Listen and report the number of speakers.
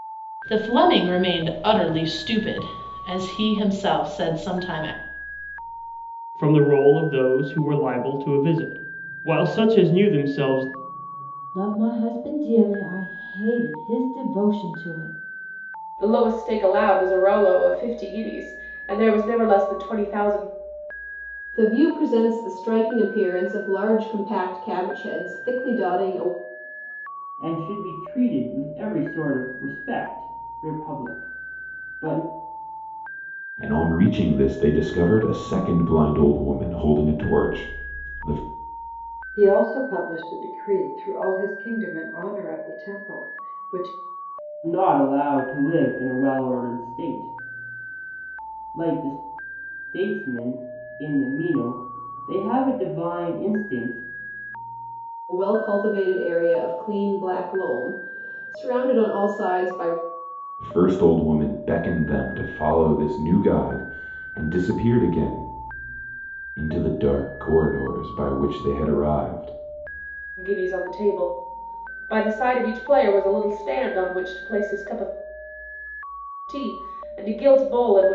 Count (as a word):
eight